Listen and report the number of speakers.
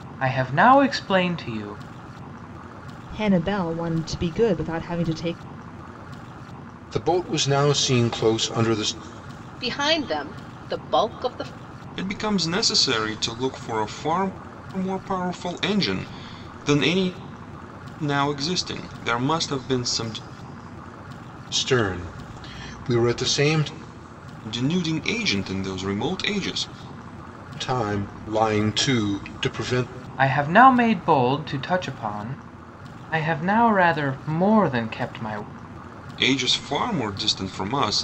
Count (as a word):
five